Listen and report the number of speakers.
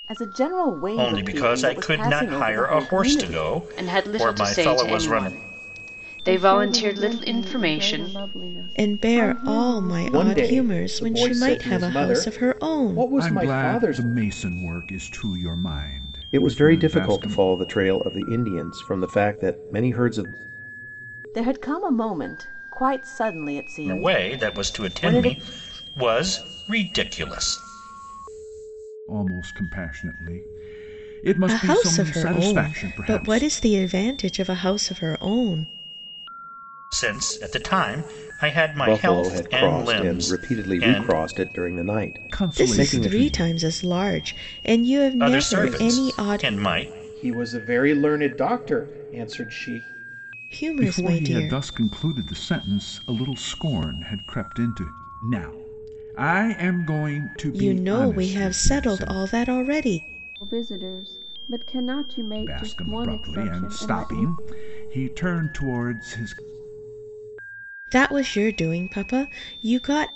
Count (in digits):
8